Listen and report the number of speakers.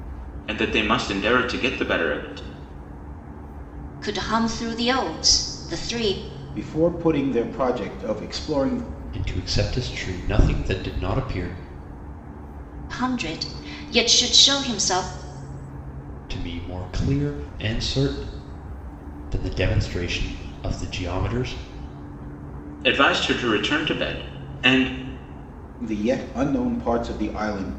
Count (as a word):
four